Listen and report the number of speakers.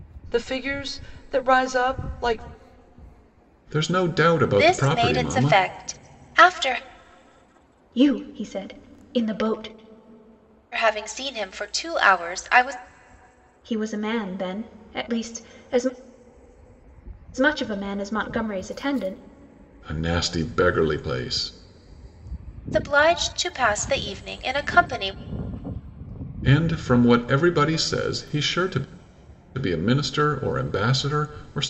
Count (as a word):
four